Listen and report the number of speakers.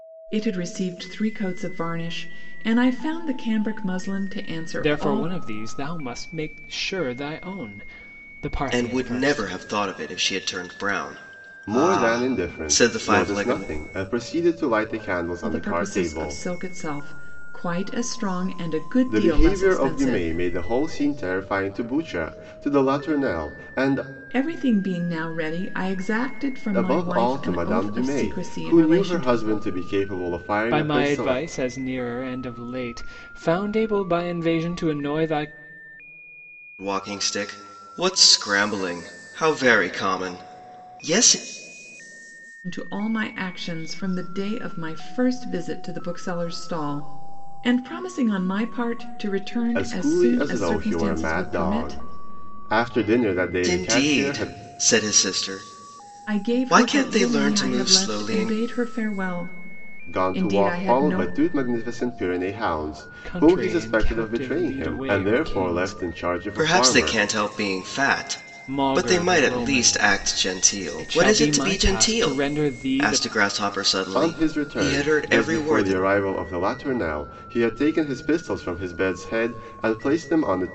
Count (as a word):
four